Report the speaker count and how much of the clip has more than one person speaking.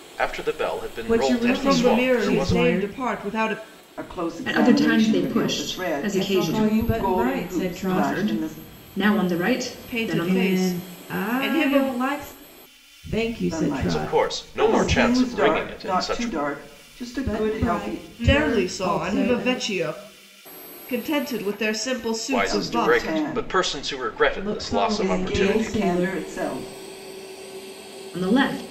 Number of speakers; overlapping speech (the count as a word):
five, about 57%